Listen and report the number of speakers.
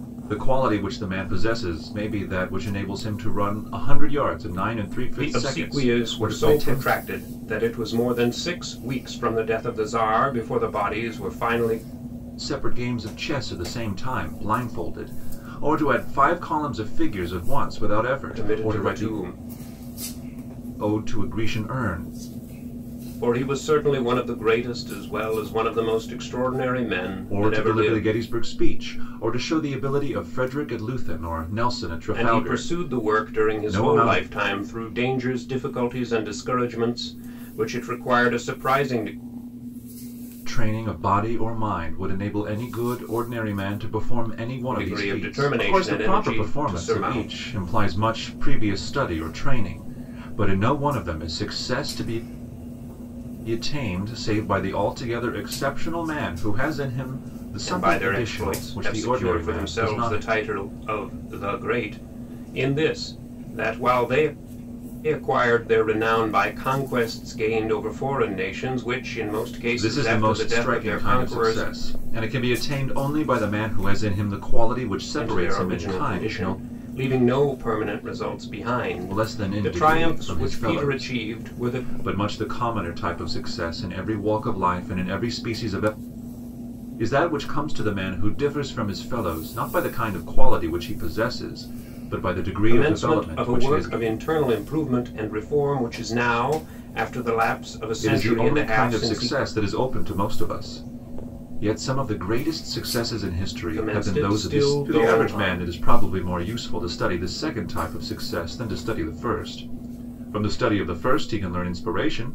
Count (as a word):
two